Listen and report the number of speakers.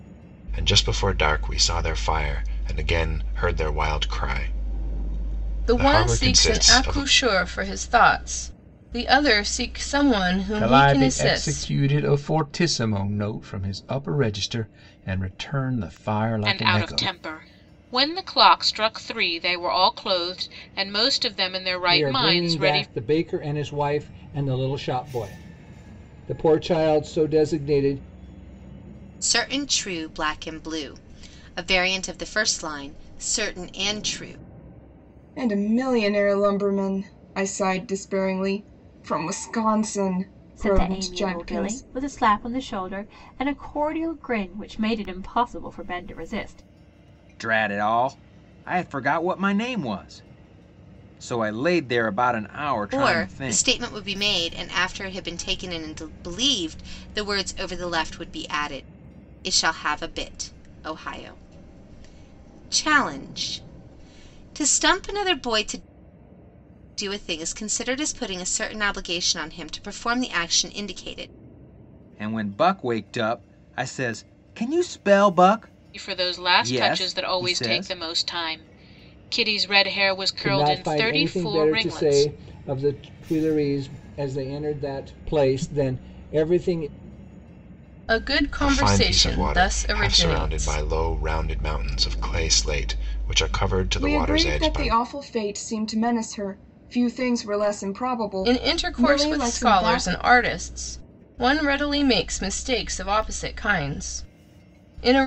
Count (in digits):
9